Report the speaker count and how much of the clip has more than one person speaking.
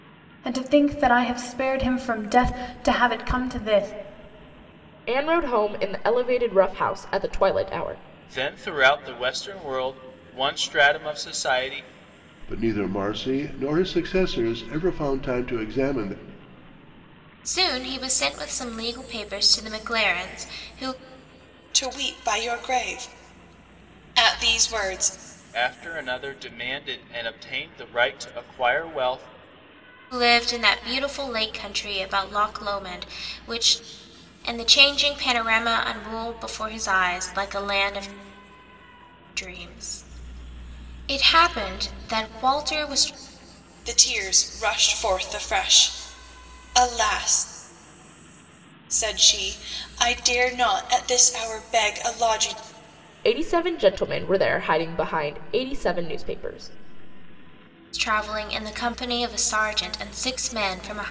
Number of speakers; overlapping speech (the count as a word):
six, no overlap